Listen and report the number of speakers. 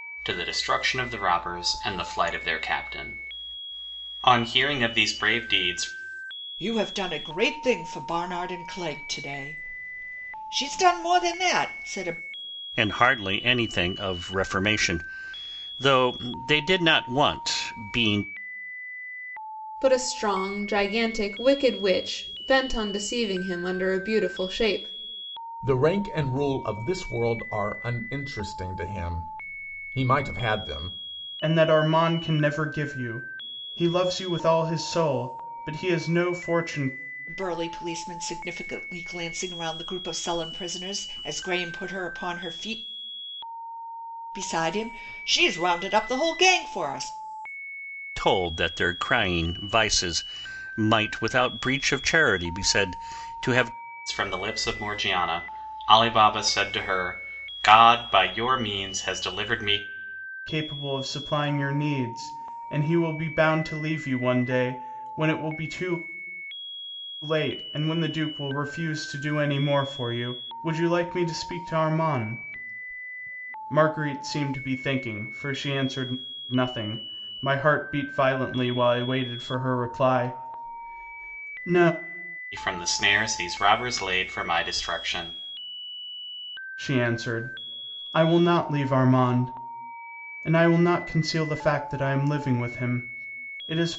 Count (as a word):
six